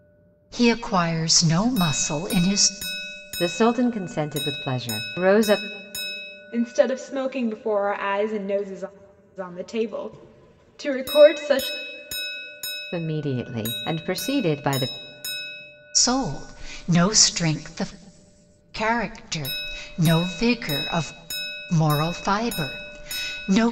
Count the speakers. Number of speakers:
3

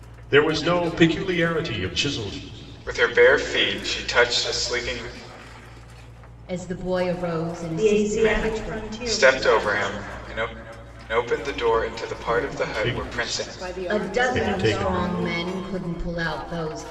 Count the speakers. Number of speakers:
4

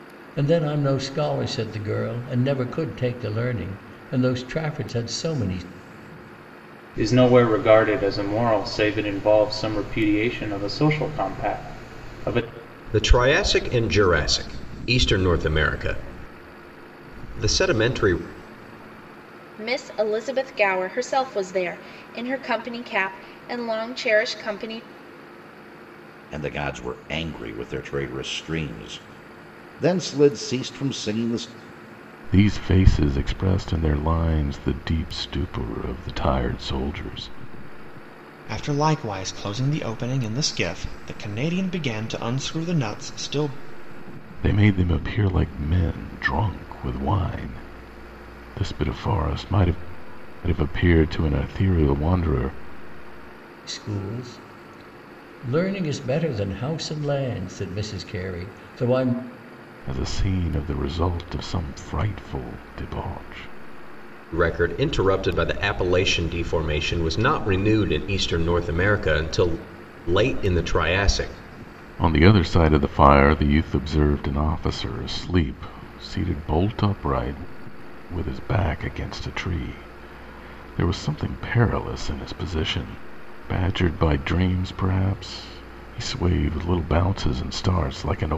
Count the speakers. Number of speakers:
7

